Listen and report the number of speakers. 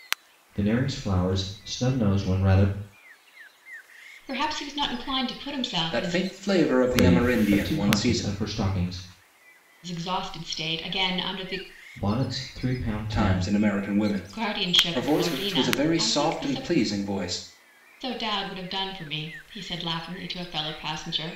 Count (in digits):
3